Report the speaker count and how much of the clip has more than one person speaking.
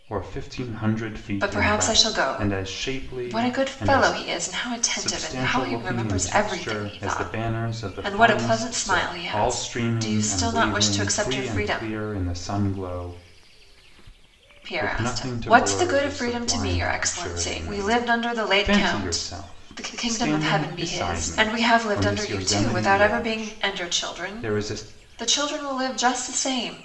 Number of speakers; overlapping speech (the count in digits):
2, about 69%